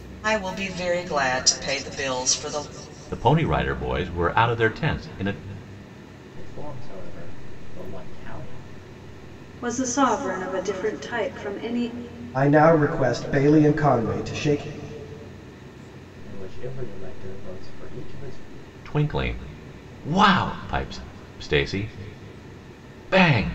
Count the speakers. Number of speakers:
5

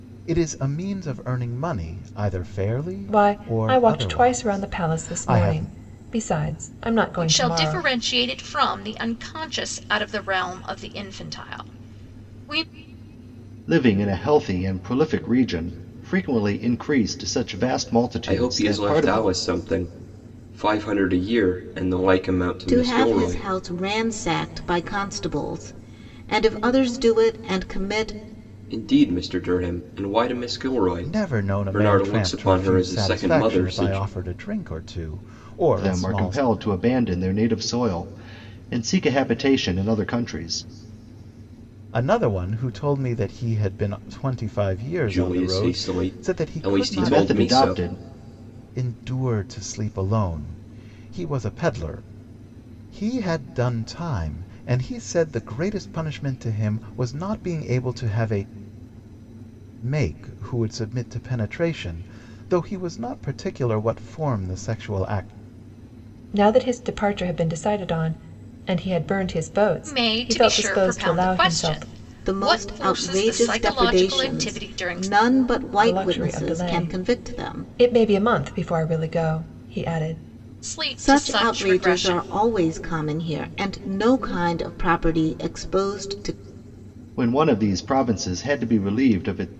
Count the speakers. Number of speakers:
6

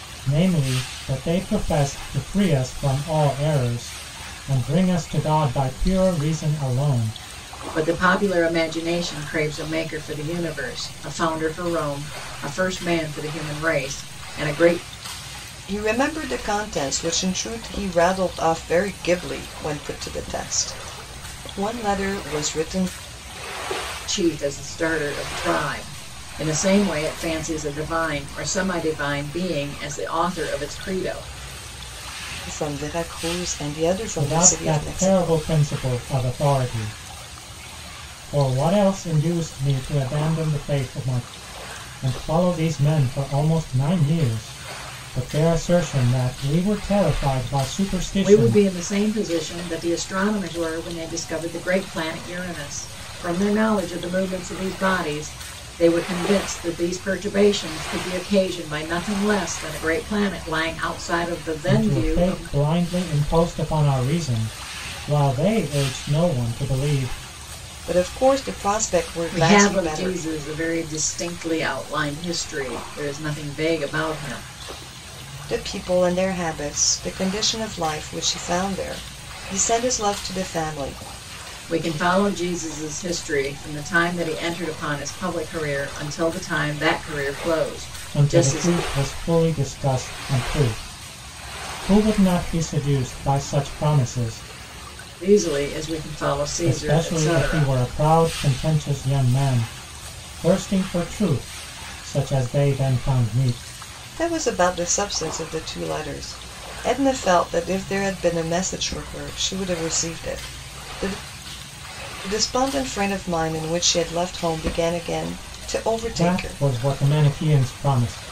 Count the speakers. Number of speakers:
3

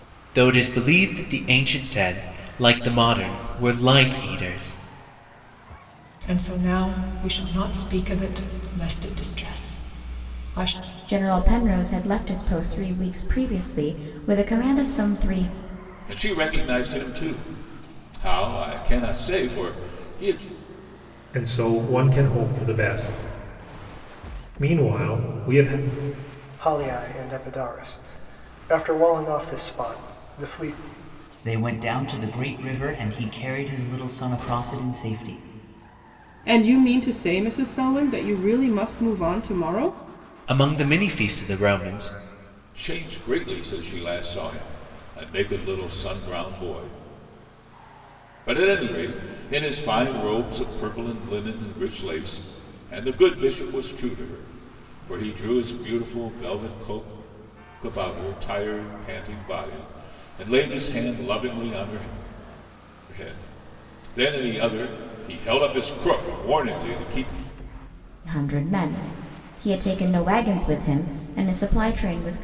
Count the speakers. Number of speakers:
8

